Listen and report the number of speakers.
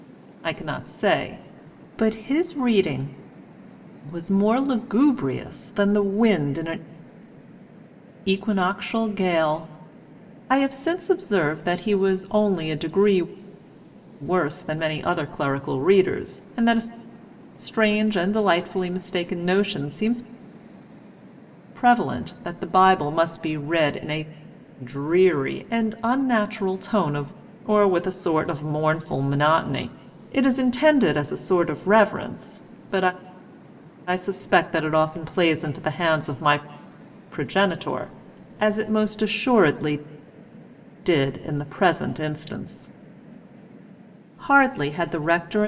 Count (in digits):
1